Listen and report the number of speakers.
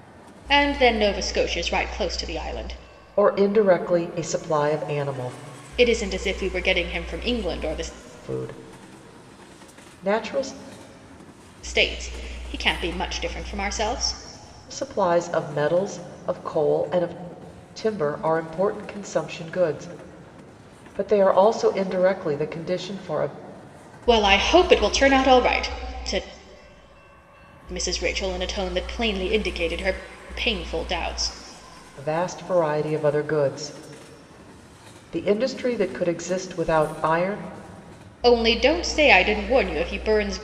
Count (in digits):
2